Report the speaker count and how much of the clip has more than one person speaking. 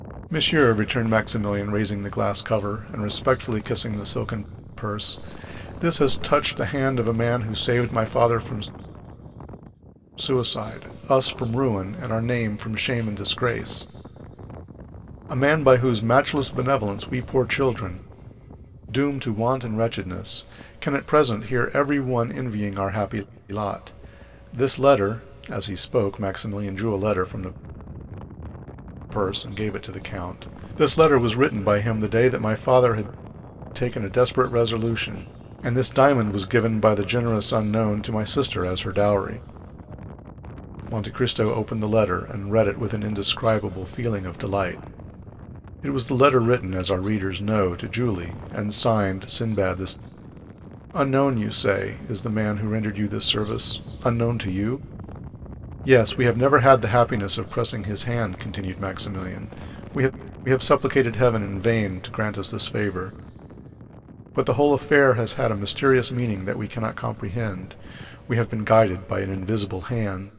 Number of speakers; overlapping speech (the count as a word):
one, no overlap